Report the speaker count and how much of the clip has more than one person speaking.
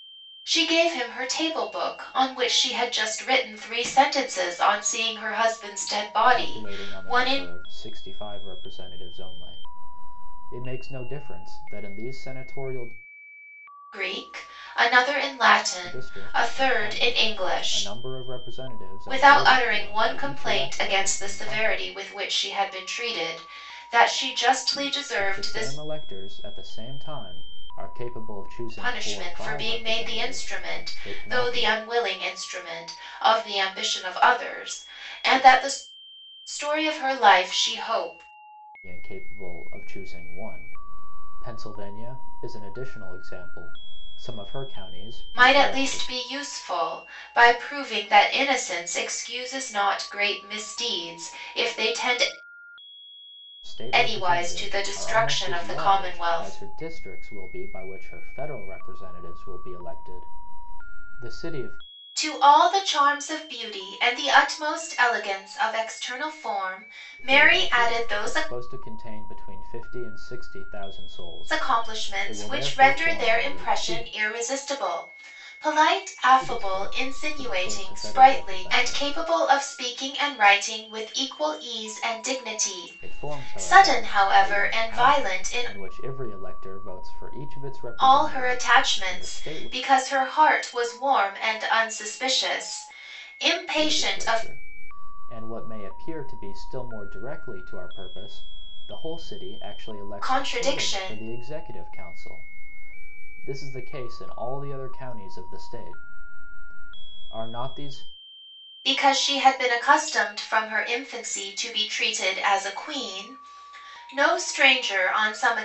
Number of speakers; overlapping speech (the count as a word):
two, about 23%